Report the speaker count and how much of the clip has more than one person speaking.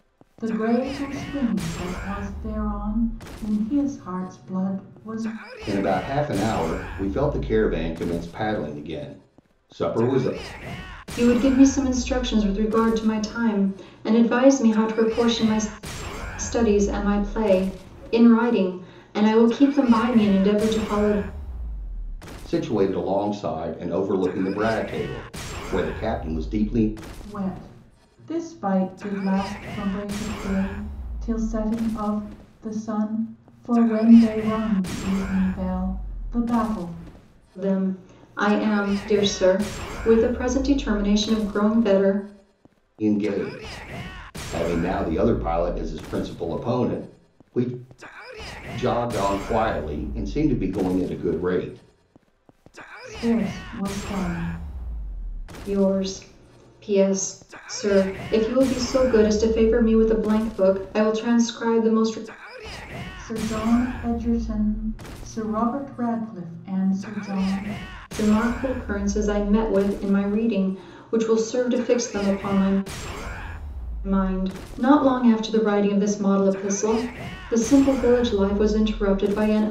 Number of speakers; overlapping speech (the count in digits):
3, no overlap